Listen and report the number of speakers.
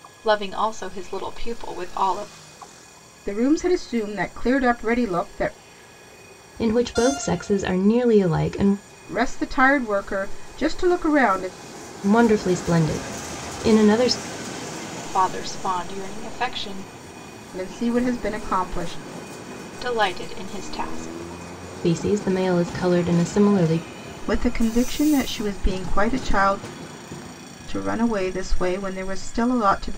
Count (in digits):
3